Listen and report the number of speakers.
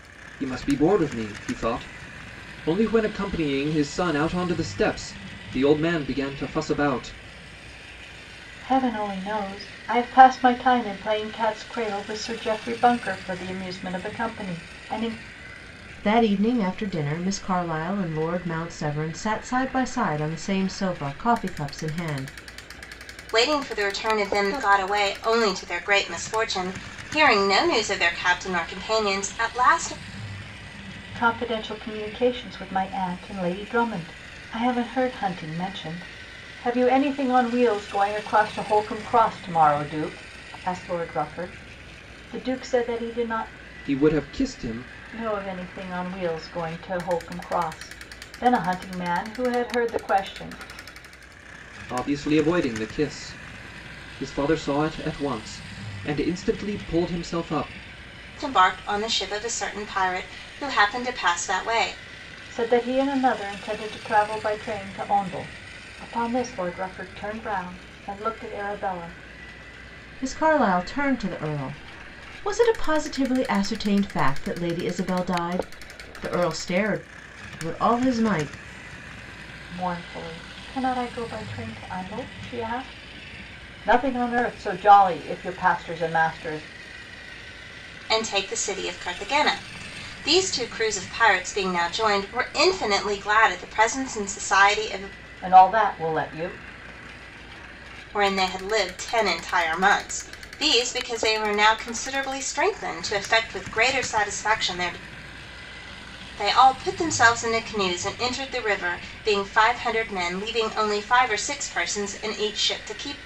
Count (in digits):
4